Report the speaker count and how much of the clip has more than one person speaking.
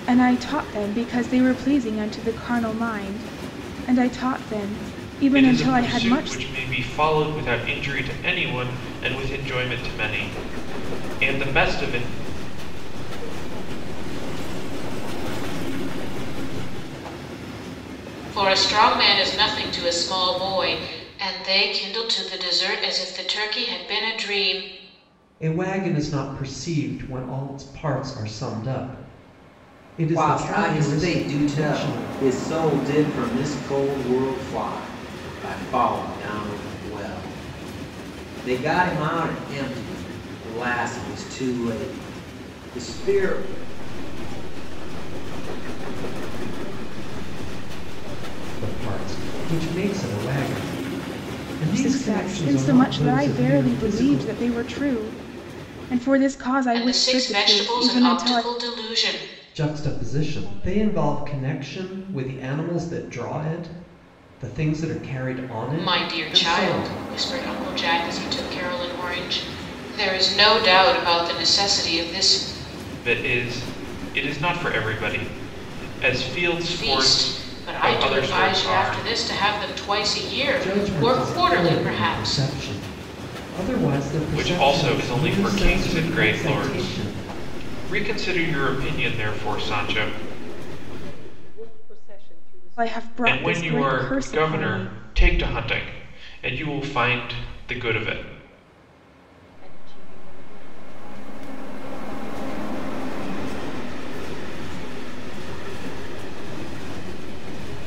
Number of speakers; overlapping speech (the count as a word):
six, about 24%